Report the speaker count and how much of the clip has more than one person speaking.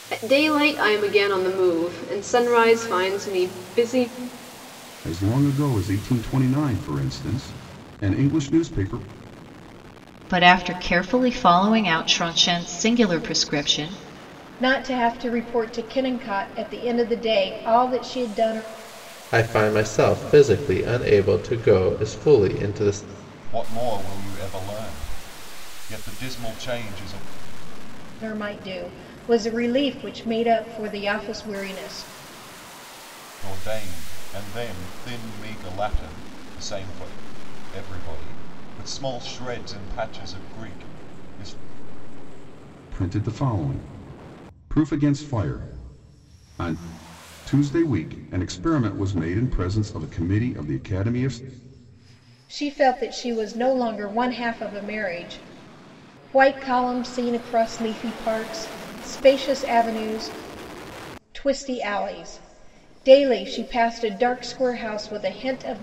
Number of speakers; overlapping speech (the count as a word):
six, no overlap